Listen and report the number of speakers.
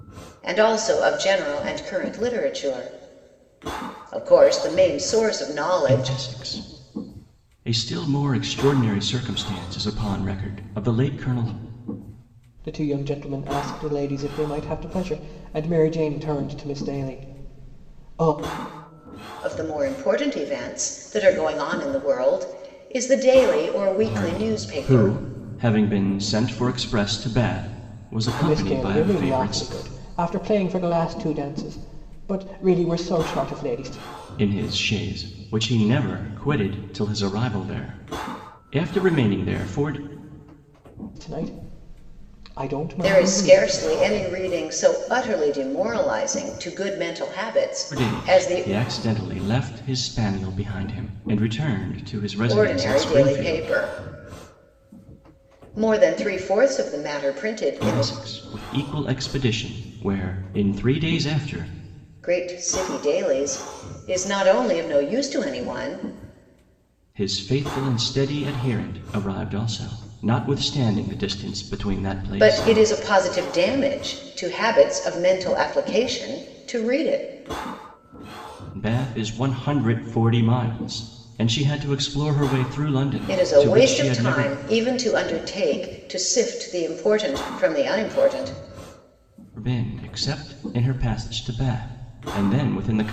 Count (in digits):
3